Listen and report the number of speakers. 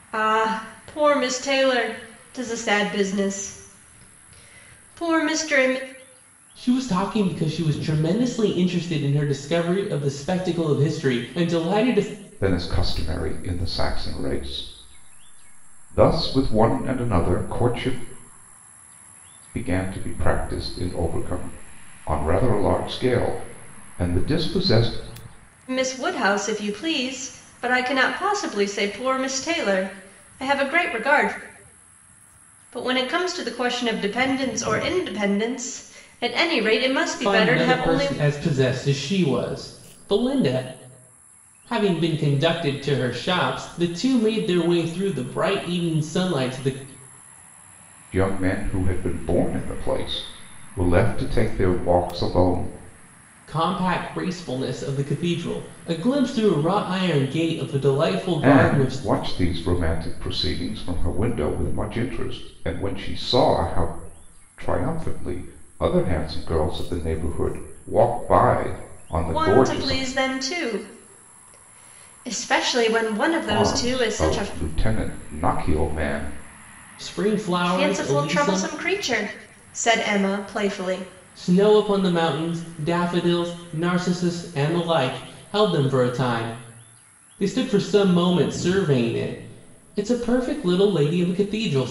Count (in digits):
3